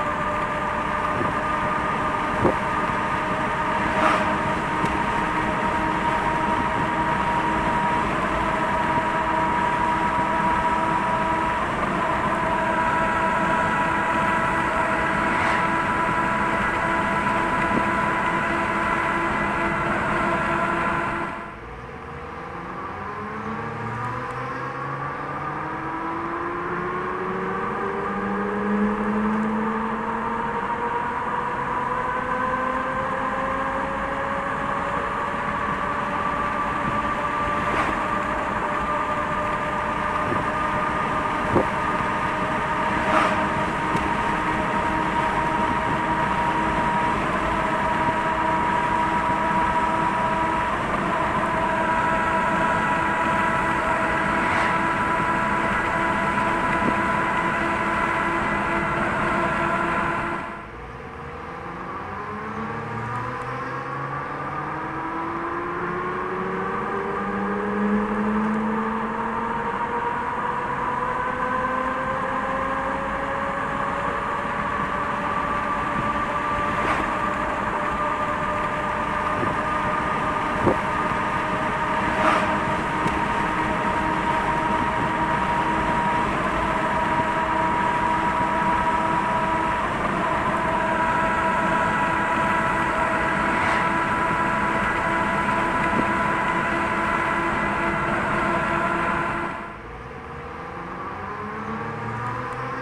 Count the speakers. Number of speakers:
0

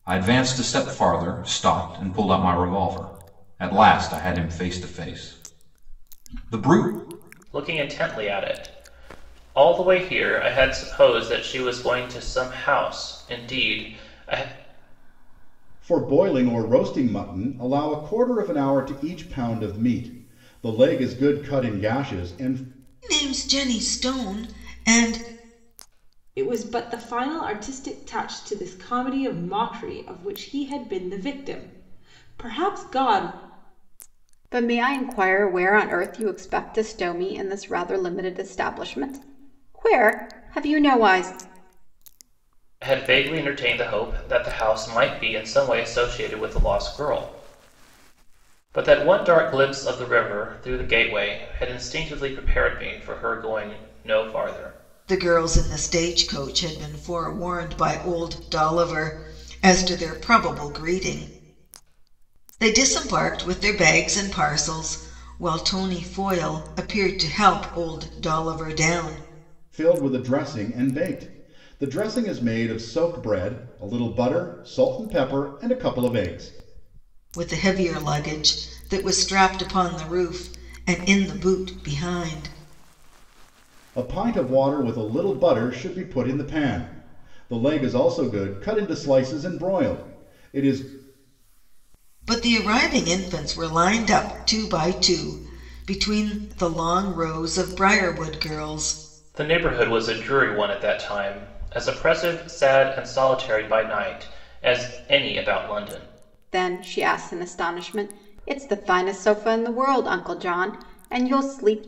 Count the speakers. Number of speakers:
6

